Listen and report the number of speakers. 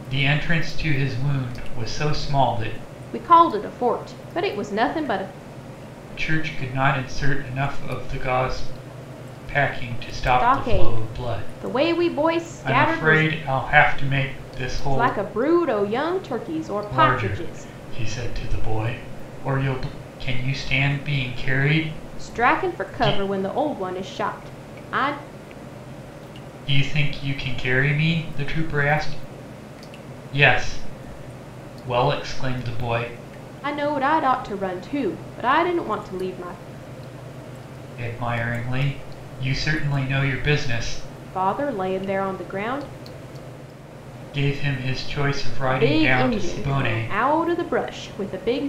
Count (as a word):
two